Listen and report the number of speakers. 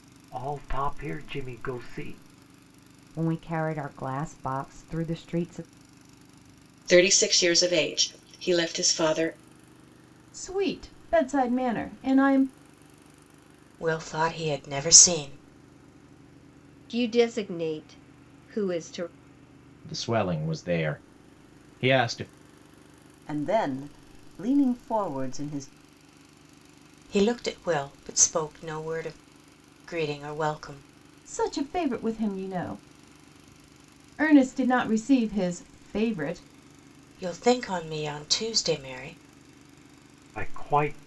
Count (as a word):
eight